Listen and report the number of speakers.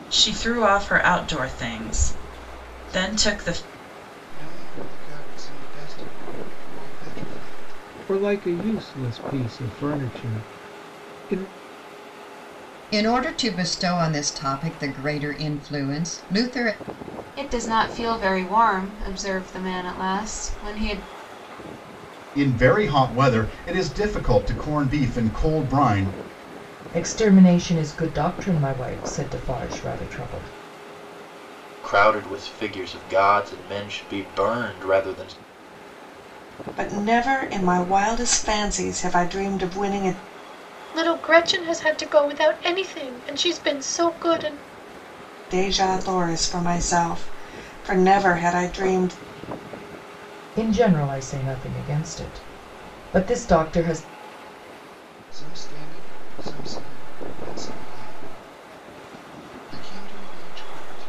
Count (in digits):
10